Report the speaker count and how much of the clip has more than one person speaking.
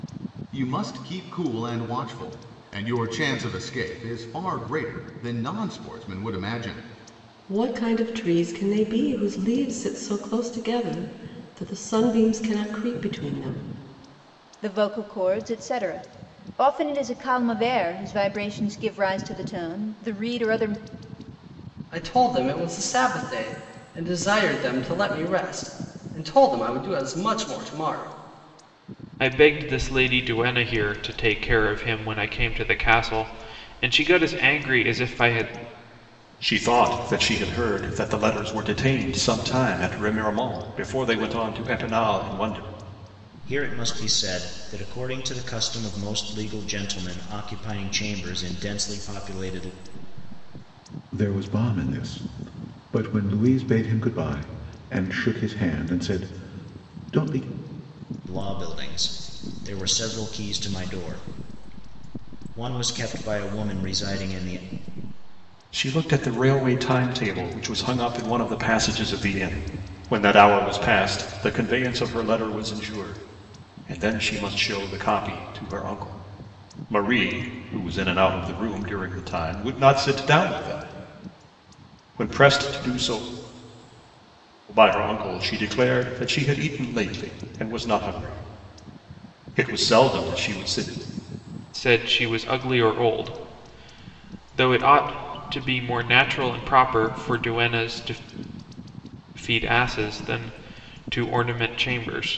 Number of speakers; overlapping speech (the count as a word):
eight, no overlap